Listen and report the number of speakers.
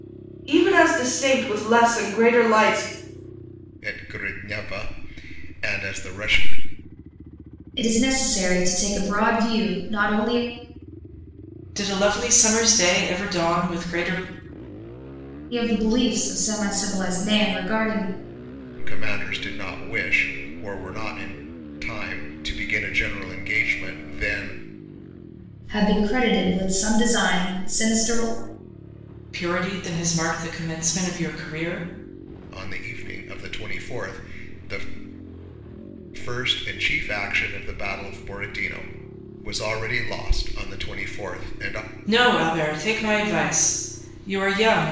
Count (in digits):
4